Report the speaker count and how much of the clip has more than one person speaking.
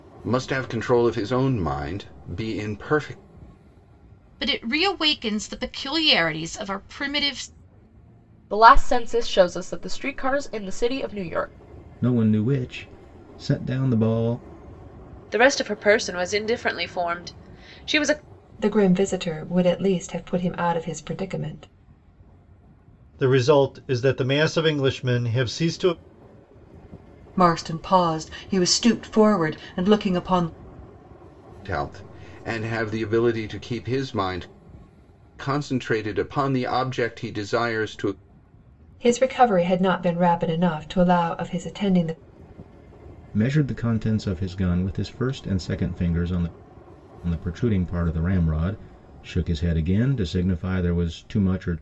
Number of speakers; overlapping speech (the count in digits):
8, no overlap